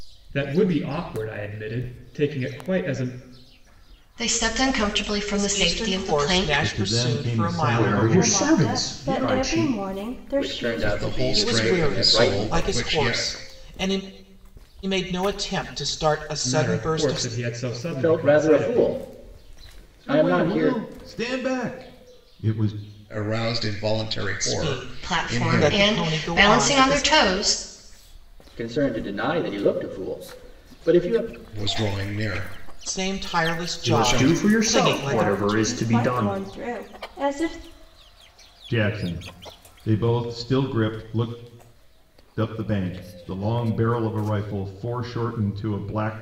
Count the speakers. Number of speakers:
8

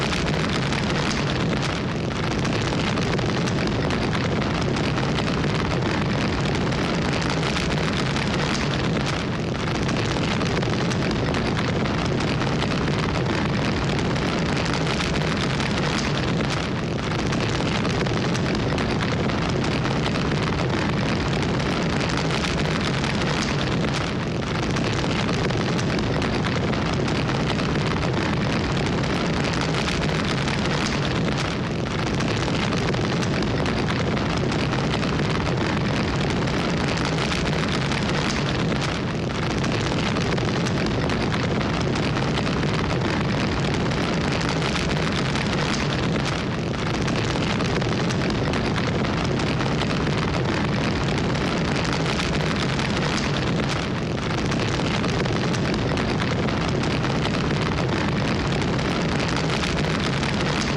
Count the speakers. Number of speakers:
0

